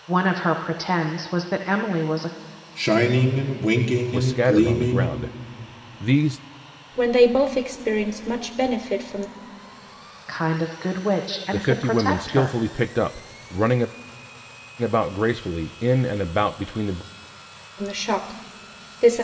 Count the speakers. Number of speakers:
4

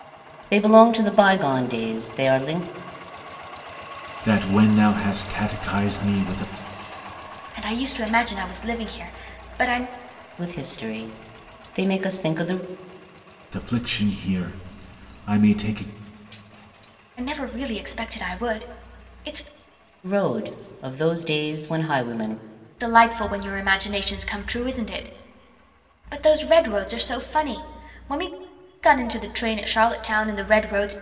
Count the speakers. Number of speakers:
3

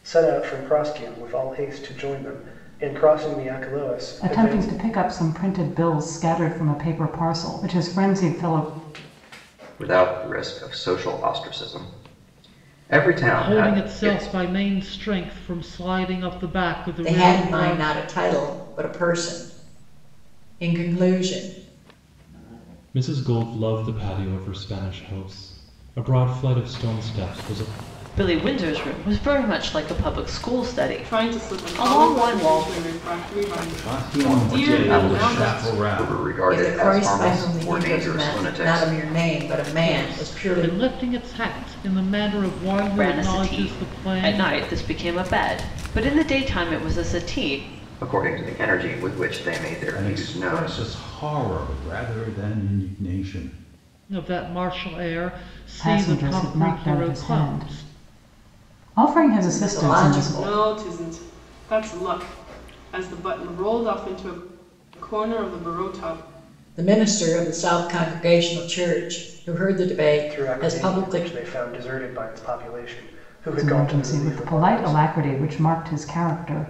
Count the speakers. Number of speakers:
9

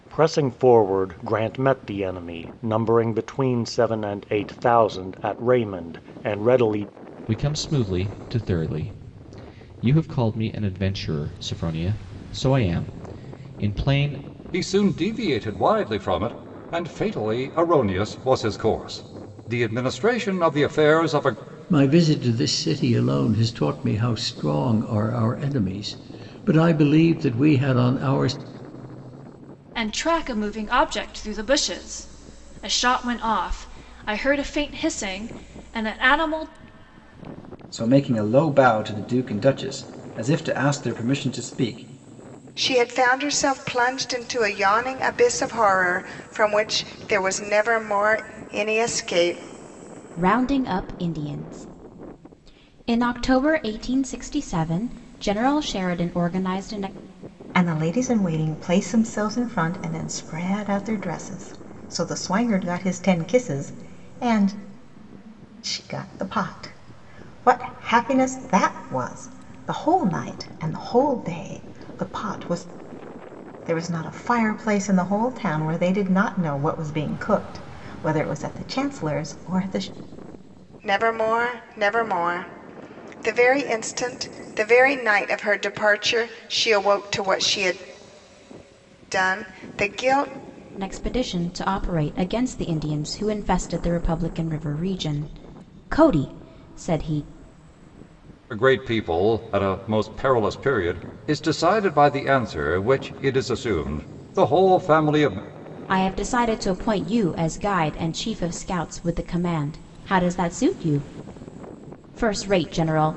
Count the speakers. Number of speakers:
9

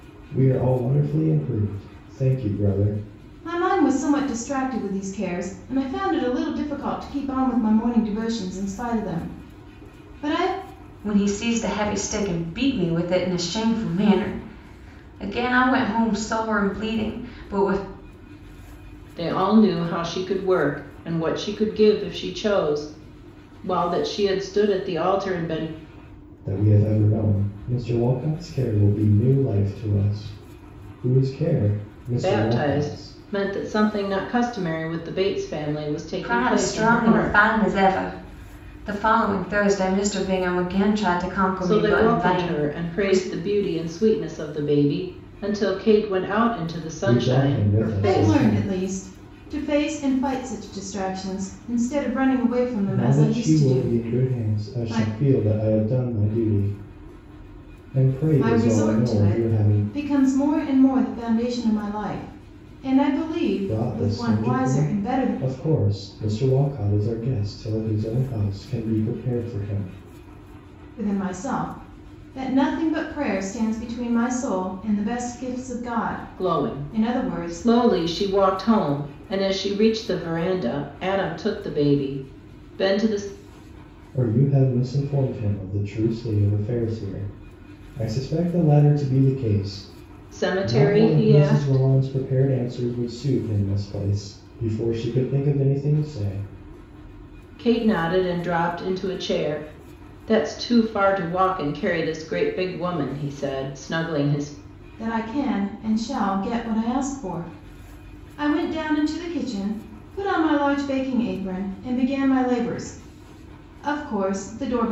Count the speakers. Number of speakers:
4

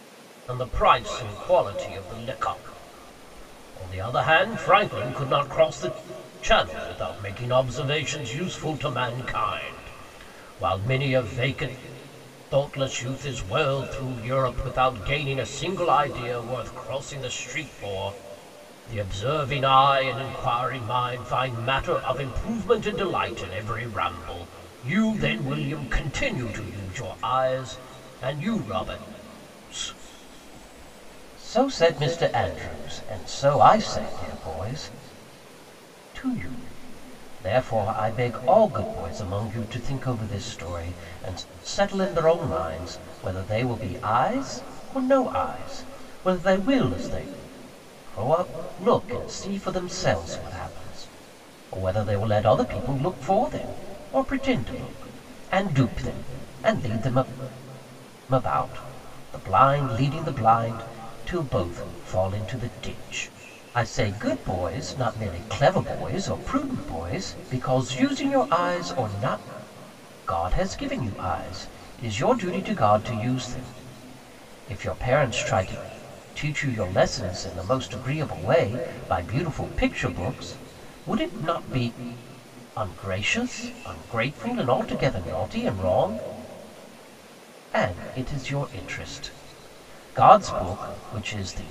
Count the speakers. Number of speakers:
1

